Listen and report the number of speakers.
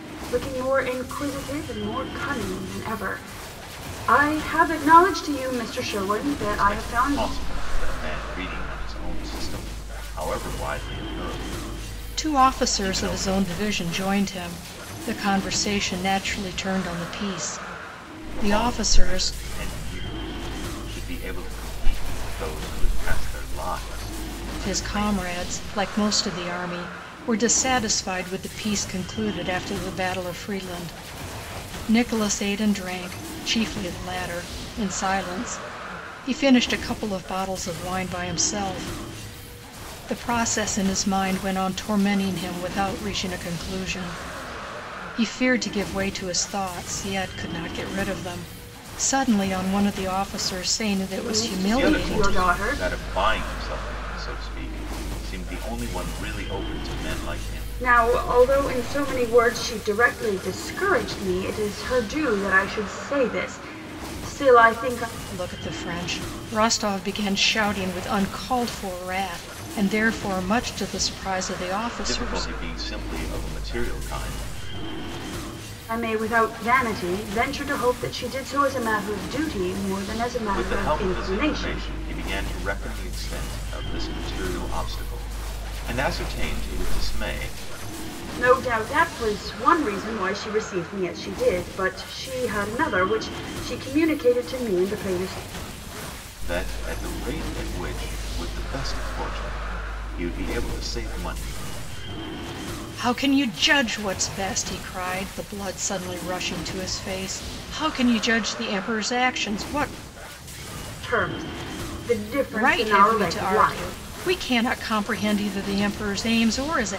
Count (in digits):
3